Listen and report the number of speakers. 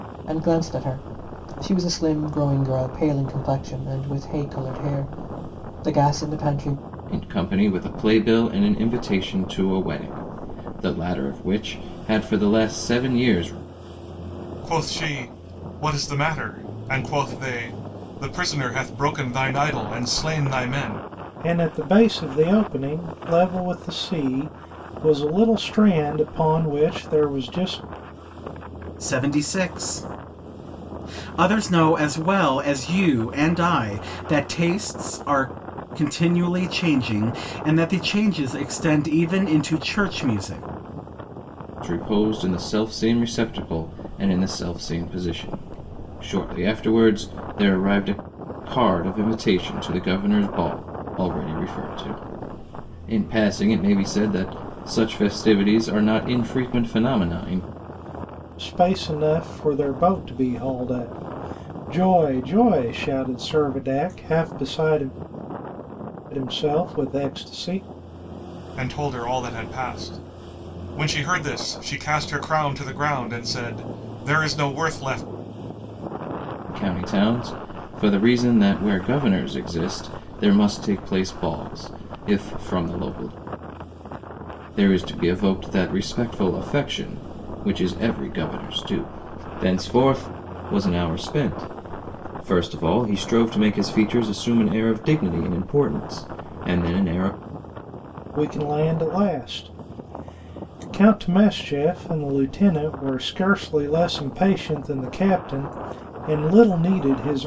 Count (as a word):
five